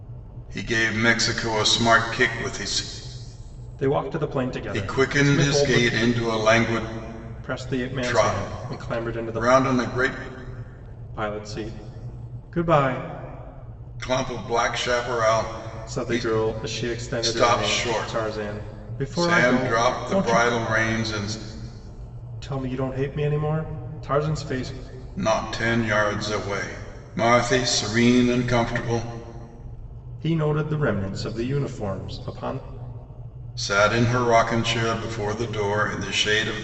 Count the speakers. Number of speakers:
2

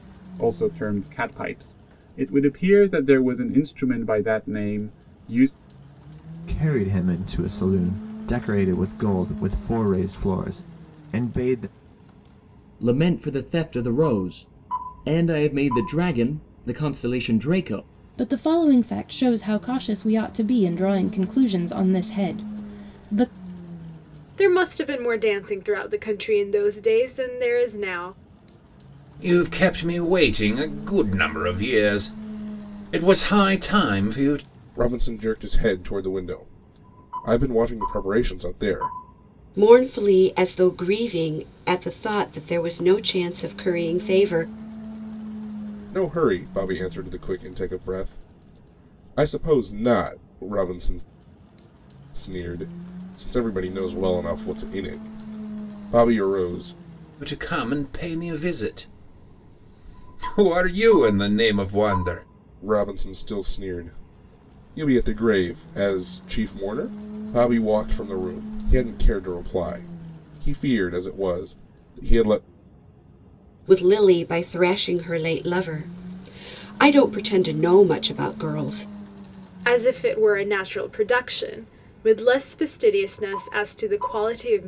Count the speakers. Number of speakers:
8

